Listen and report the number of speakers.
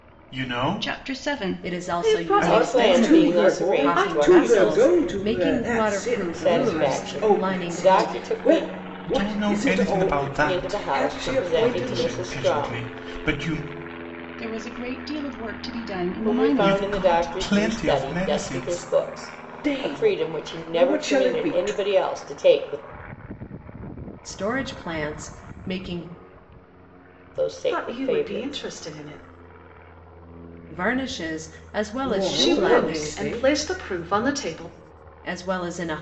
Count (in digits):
6